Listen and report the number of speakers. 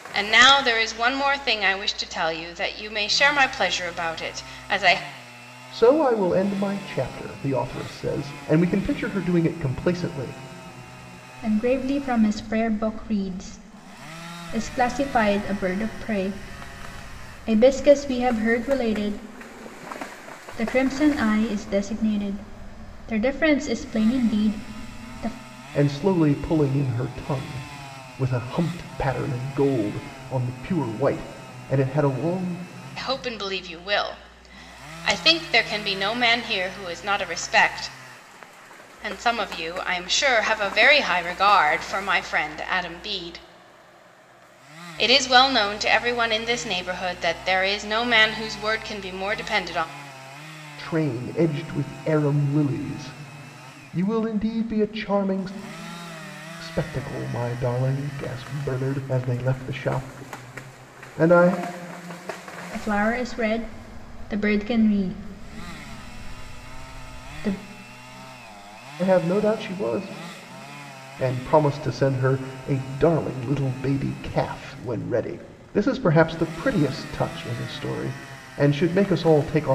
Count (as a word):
three